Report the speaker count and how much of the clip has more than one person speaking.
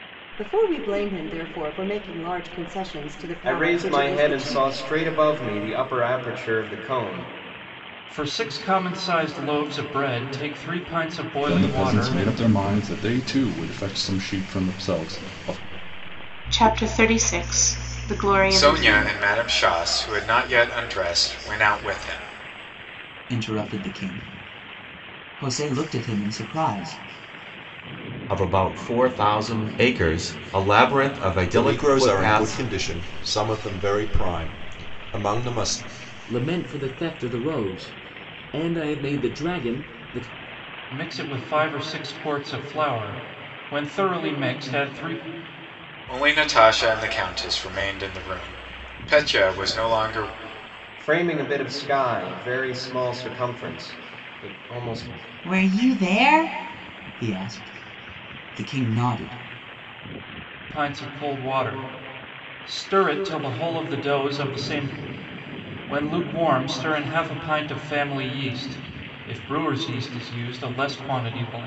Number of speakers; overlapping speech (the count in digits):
10, about 6%